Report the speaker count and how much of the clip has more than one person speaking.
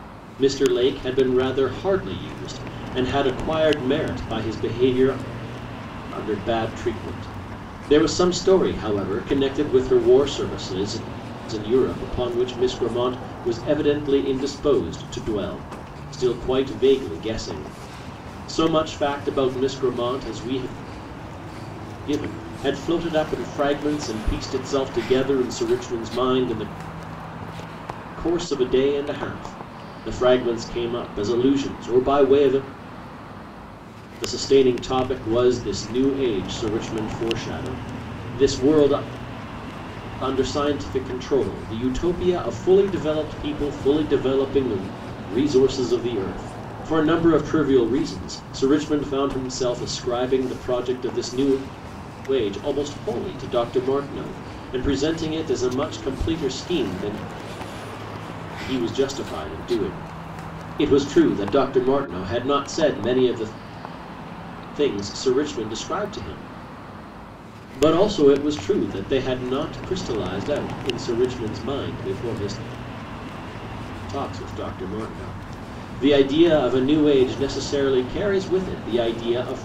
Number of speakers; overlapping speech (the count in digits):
1, no overlap